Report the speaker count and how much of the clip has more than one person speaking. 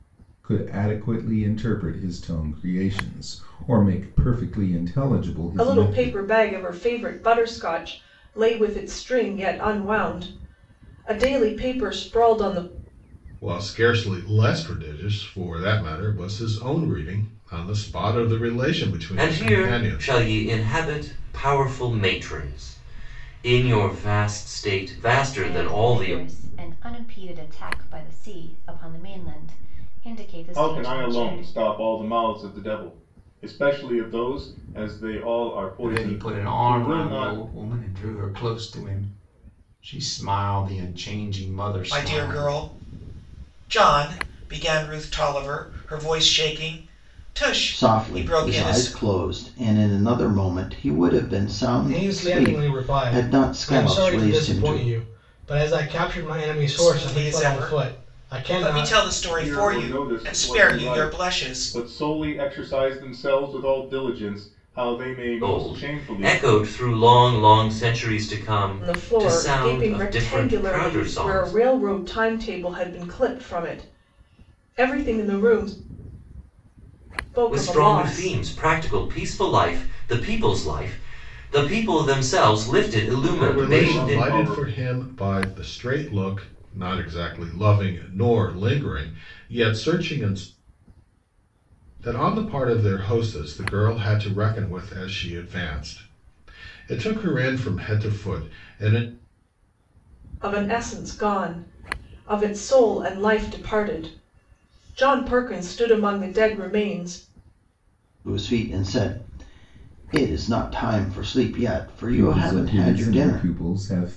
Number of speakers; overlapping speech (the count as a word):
ten, about 20%